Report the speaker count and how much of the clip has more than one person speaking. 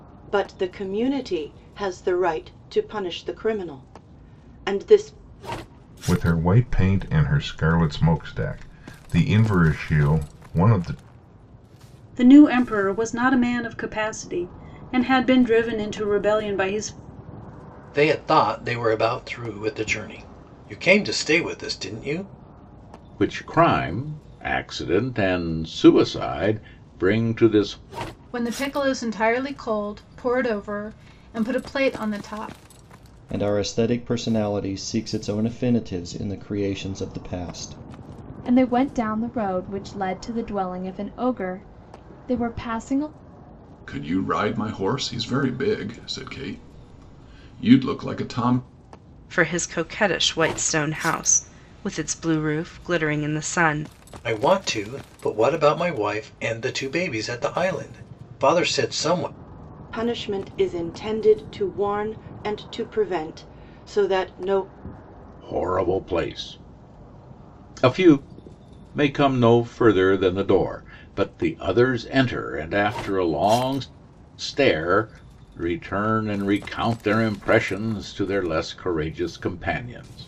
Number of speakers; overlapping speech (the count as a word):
ten, no overlap